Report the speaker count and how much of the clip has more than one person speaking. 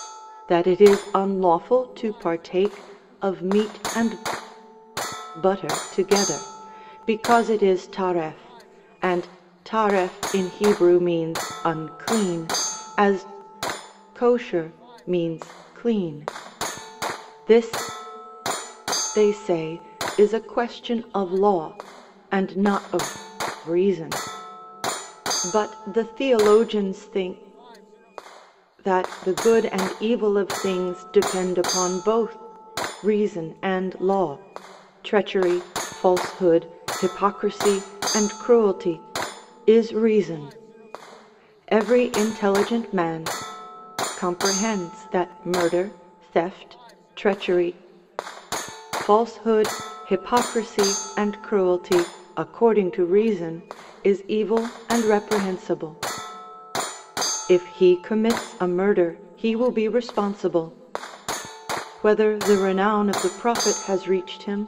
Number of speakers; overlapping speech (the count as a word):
one, no overlap